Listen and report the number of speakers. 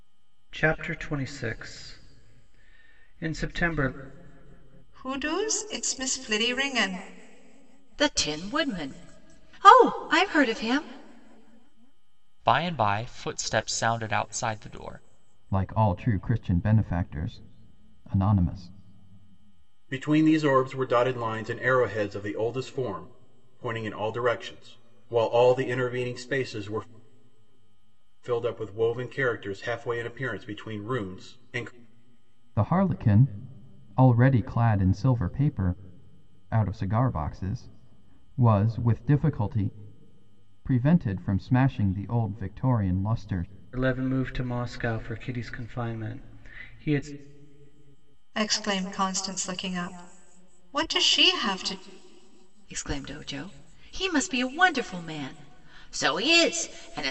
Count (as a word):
six